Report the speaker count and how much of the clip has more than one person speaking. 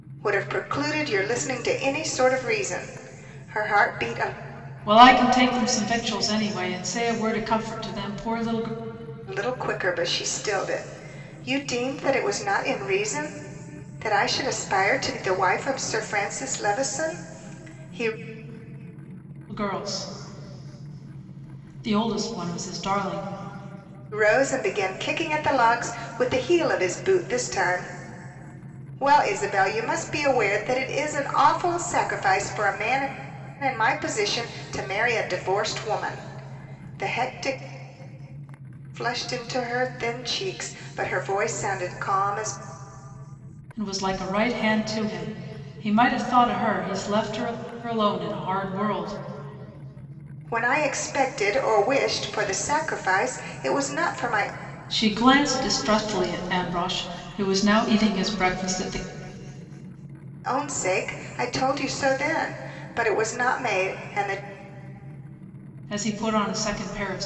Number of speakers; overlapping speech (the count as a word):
two, no overlap